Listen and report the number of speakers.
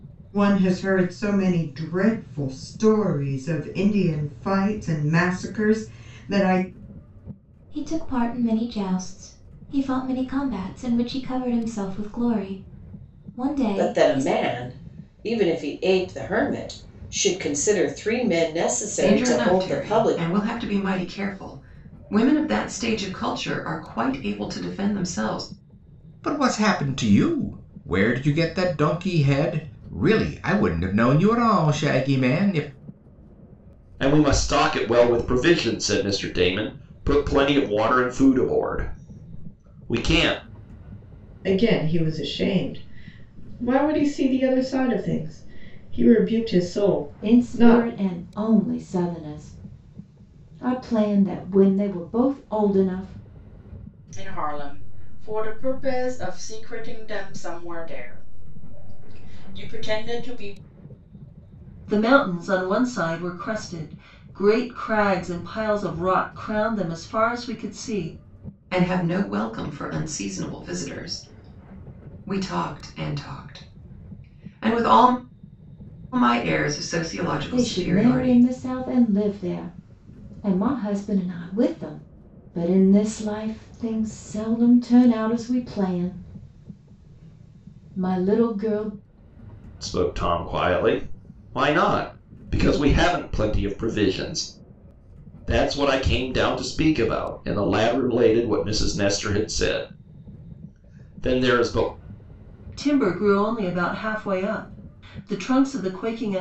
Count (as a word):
ten